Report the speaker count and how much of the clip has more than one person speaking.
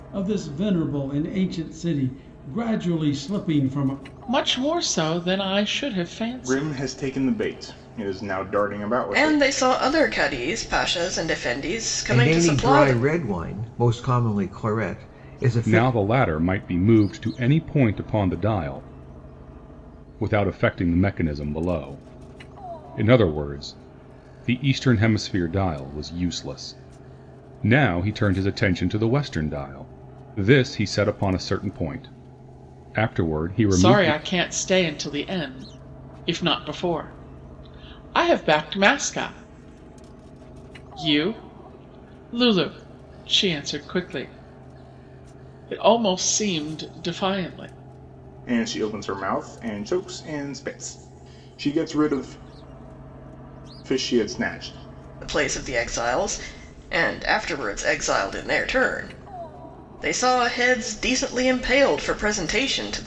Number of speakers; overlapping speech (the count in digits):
6, about 4%